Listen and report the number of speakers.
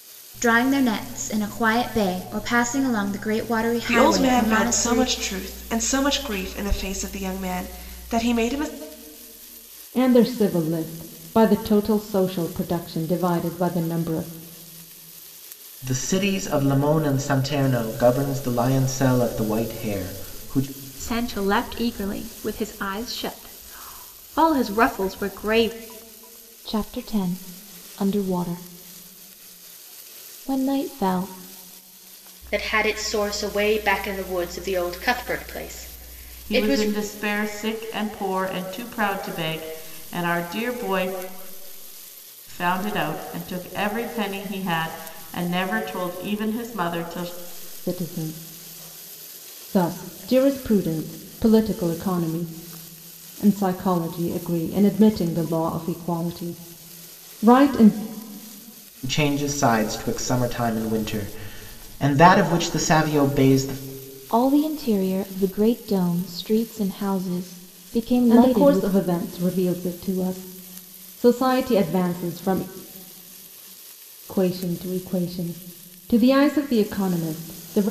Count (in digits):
8